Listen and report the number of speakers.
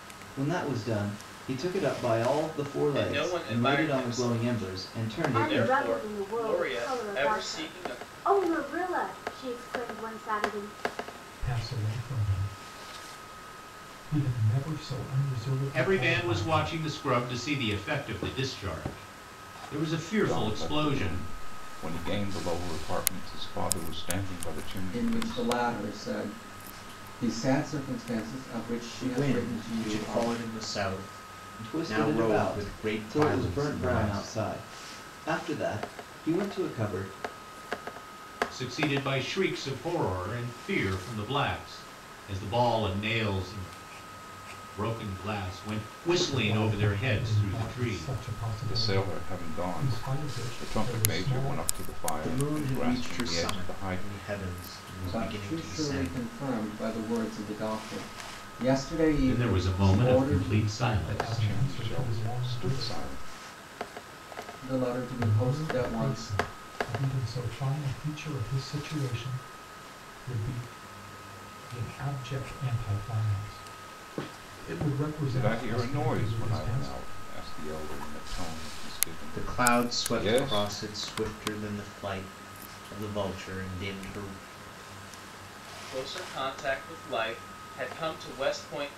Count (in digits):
8